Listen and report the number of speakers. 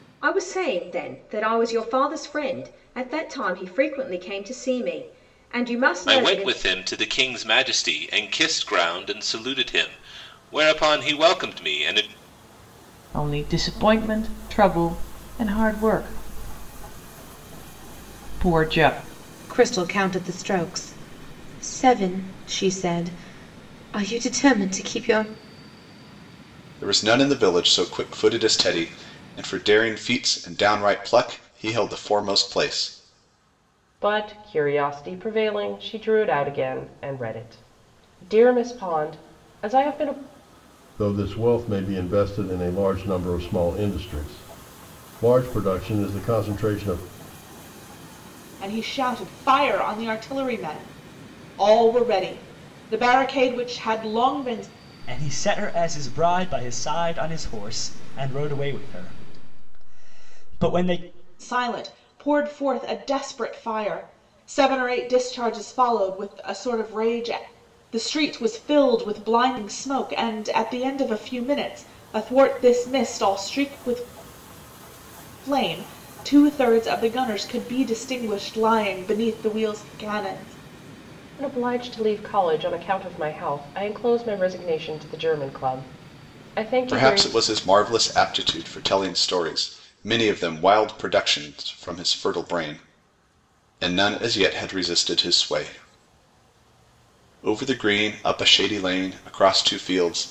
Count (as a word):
nine